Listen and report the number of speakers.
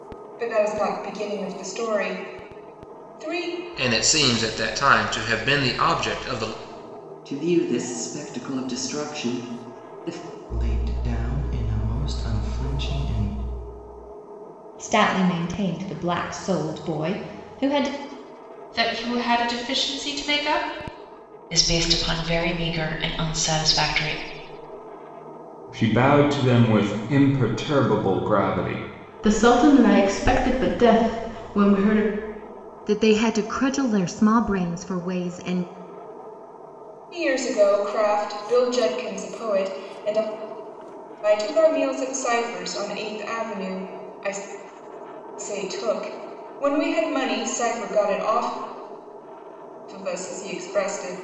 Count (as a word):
ten